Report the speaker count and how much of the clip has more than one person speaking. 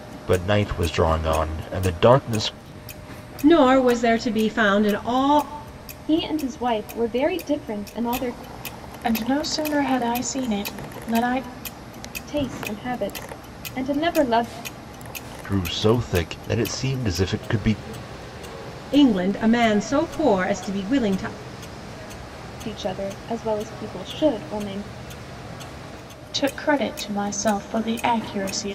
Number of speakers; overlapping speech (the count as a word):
four, no overlap